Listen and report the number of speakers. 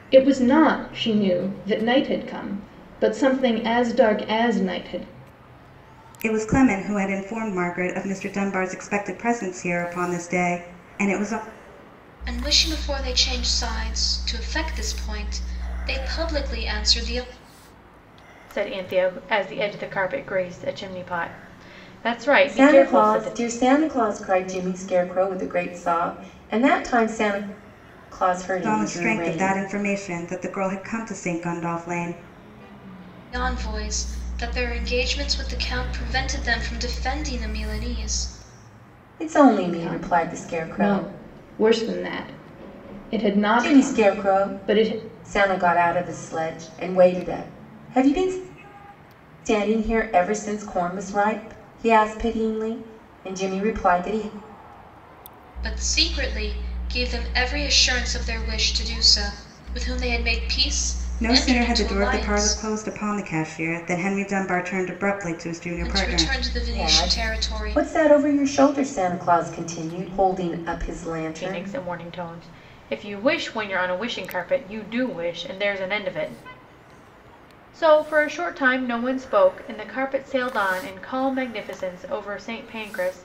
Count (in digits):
5